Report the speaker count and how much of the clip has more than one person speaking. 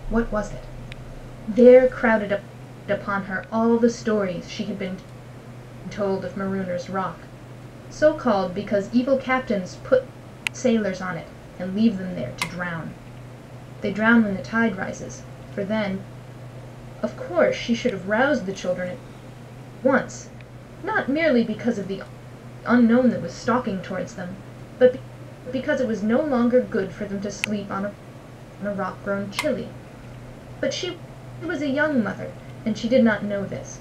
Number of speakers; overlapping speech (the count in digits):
1, no overlap